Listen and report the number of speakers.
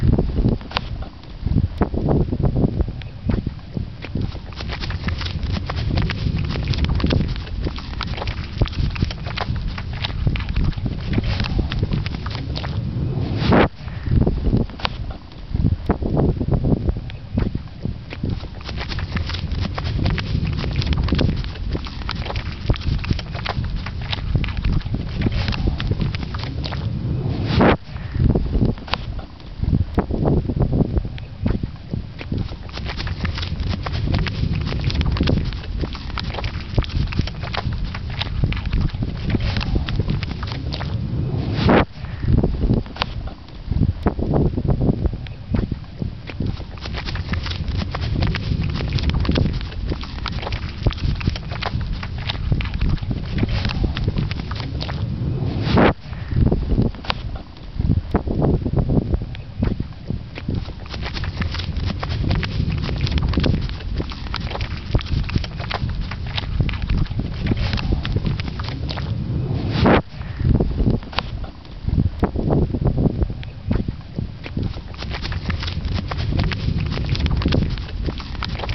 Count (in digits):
0